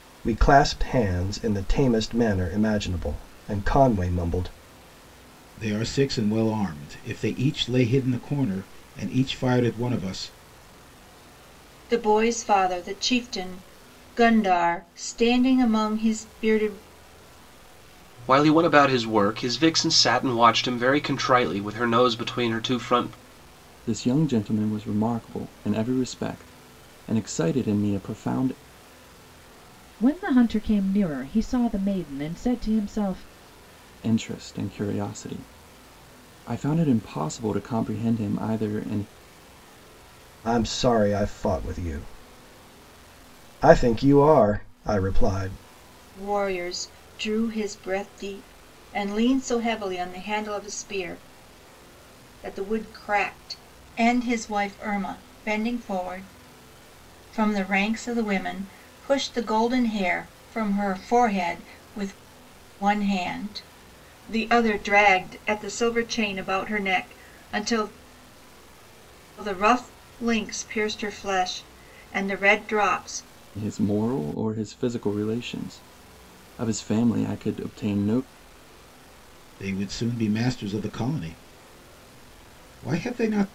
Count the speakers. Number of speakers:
6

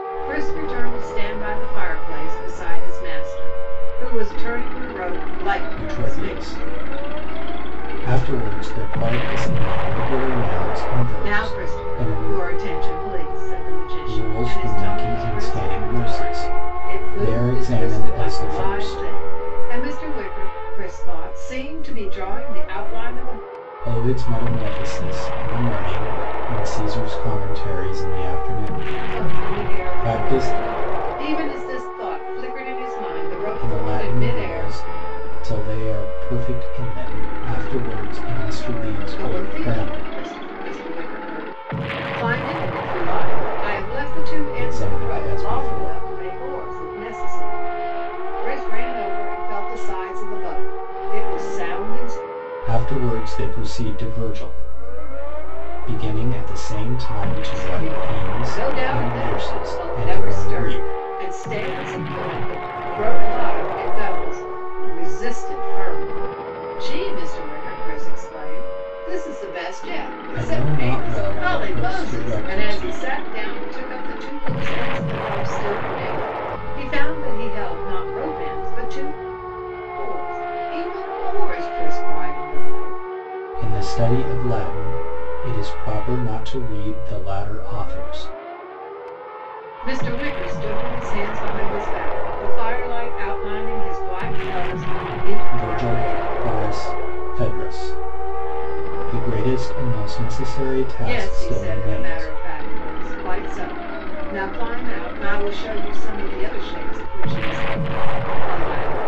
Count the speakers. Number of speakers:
2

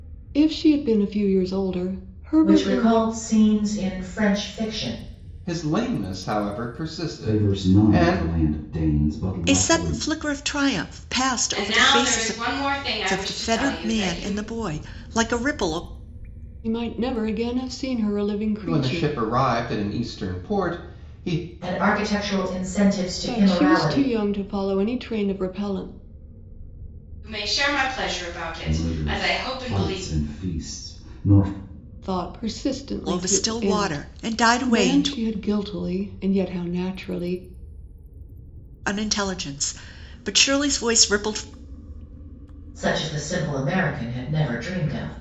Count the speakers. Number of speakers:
6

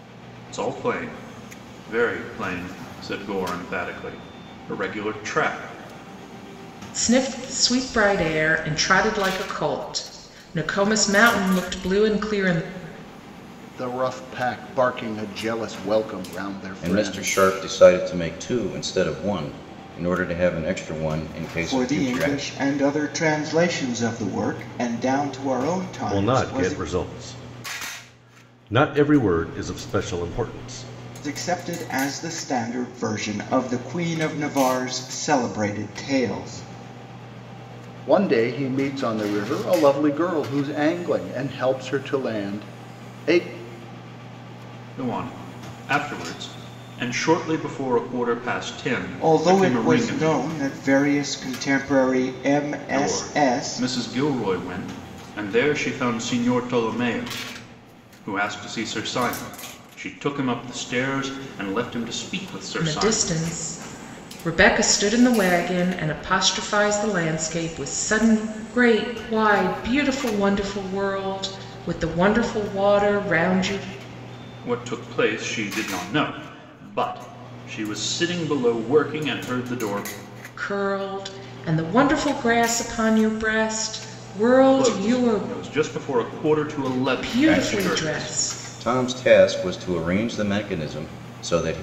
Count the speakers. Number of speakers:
6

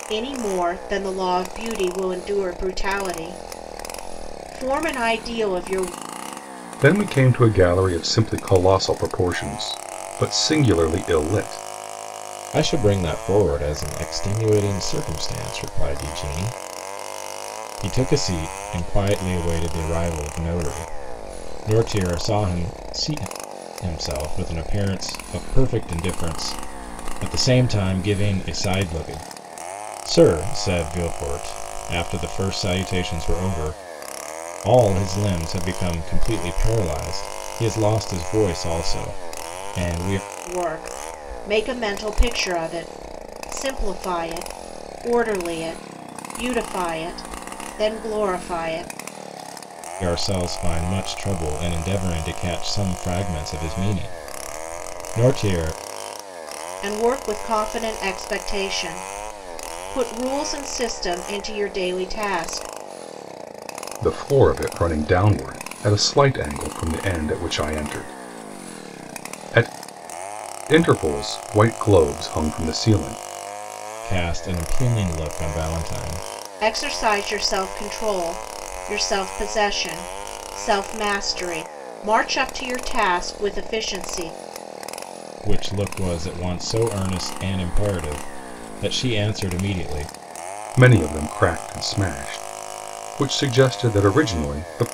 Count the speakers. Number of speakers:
3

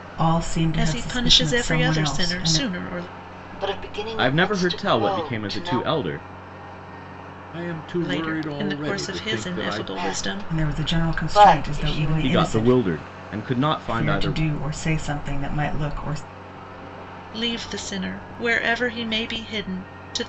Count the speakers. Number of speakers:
5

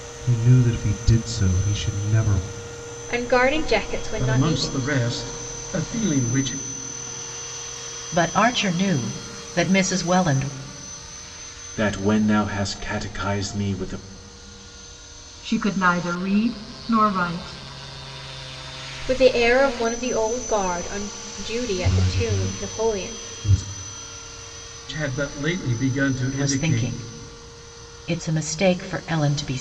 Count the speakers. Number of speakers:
6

